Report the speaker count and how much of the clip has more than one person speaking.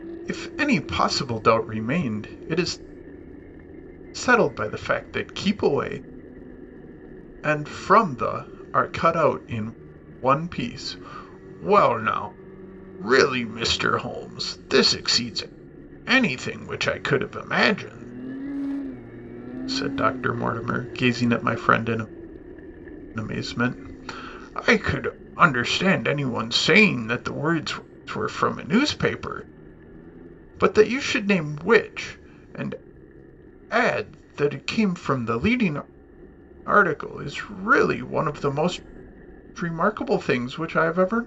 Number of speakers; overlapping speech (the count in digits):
1, no overlap